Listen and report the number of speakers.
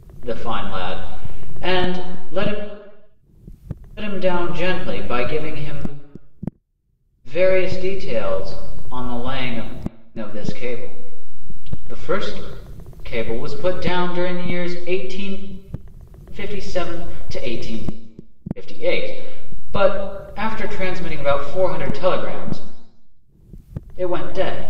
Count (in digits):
1